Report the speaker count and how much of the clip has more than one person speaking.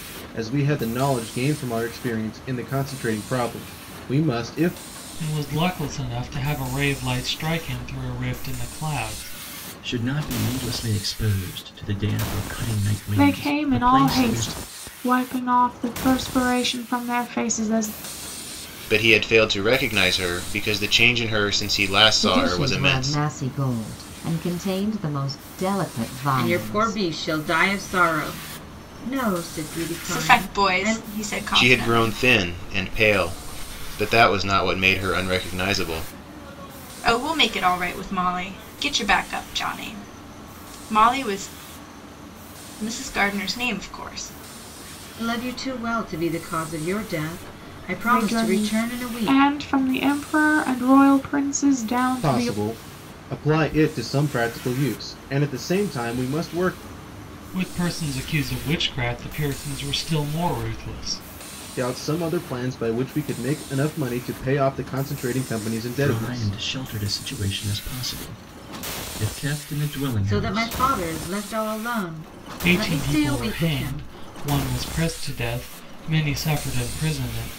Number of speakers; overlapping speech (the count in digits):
8, about 12%